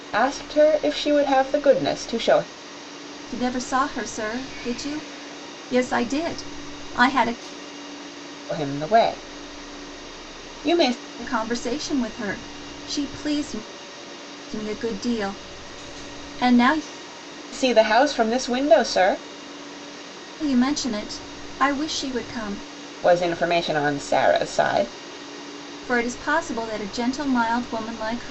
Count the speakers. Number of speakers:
2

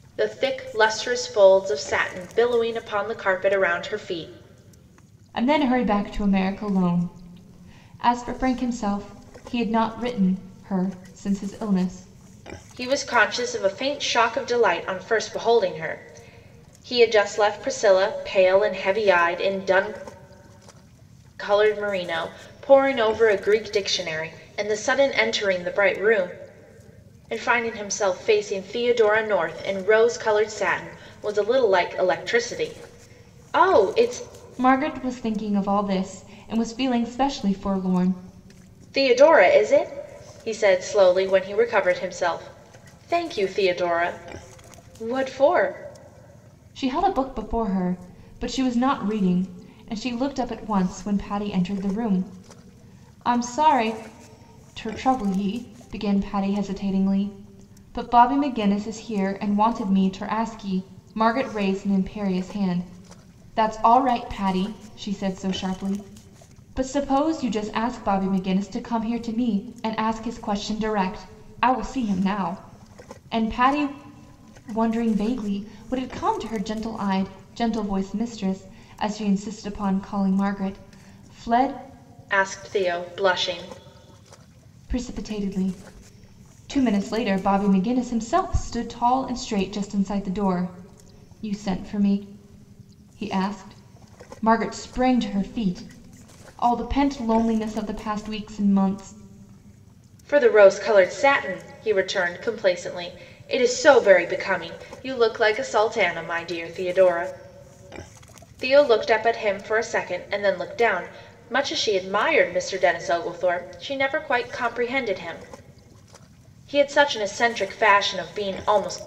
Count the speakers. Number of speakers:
2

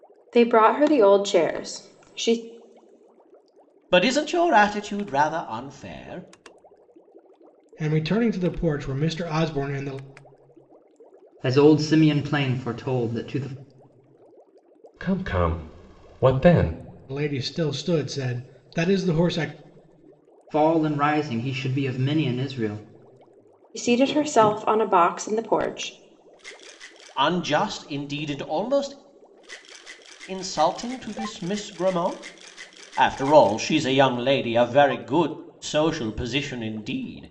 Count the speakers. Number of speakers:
5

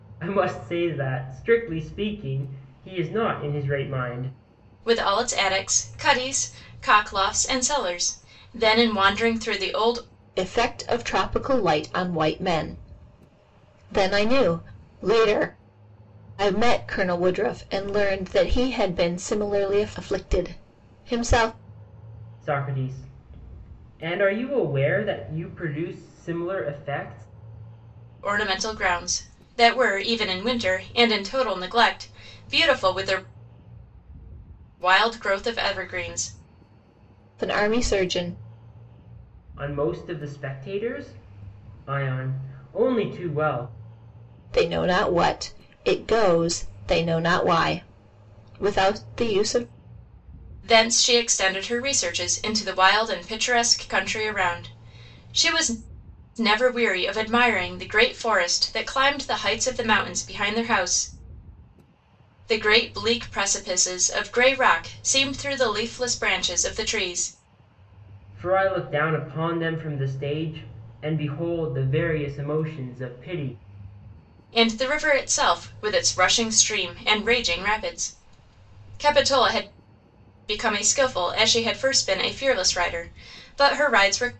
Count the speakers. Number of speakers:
3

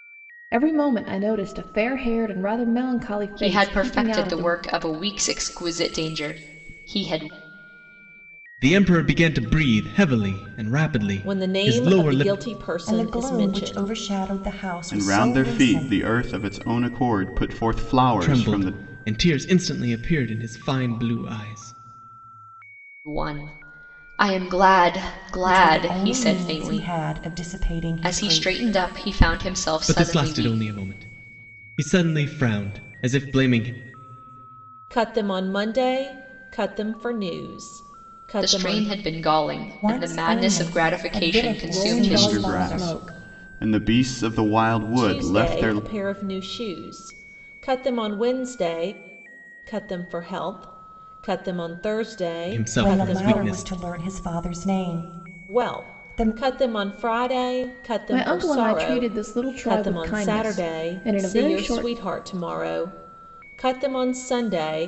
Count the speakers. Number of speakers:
6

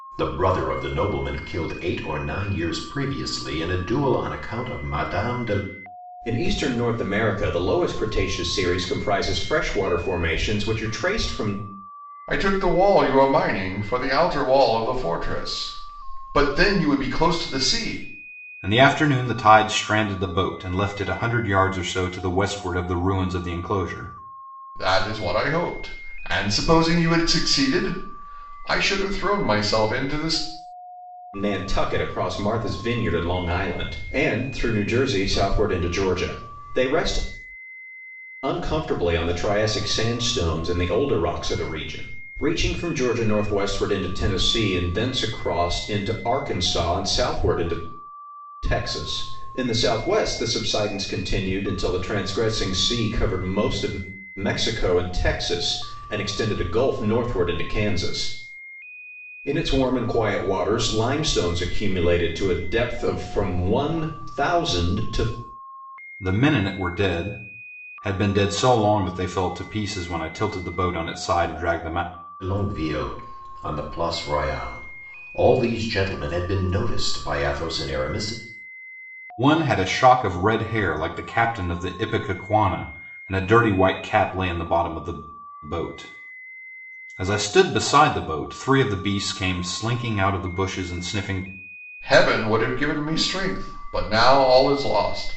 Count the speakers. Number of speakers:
4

